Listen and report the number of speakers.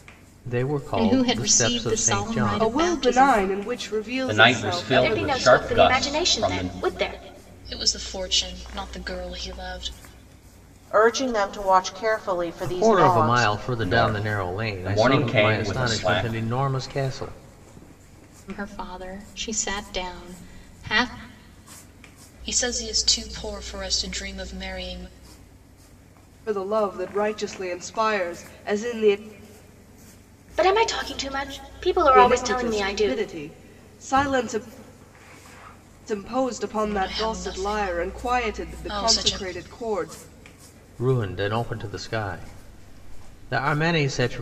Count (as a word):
seven